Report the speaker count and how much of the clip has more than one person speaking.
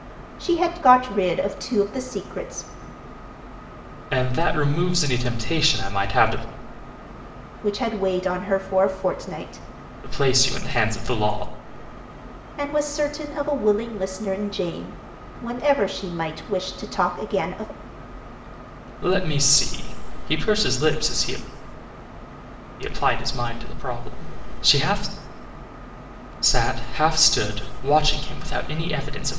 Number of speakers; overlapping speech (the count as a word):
two, no overlap